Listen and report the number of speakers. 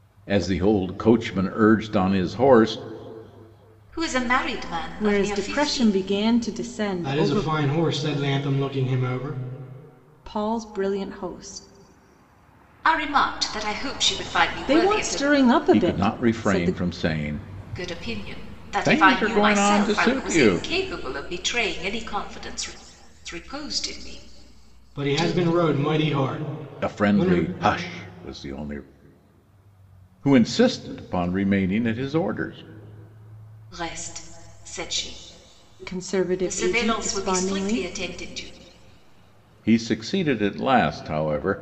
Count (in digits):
4